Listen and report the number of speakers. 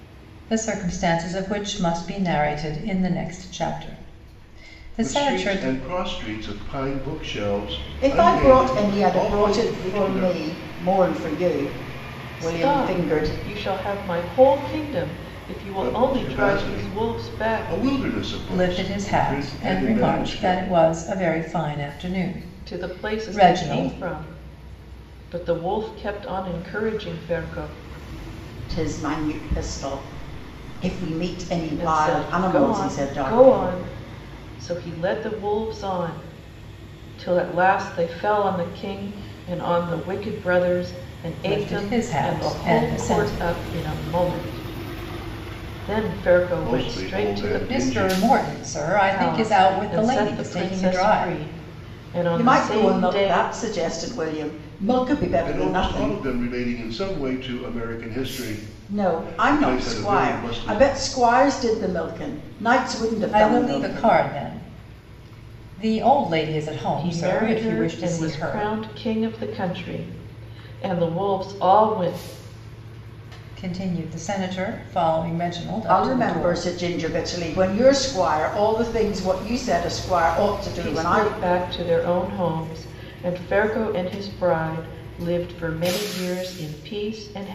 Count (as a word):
four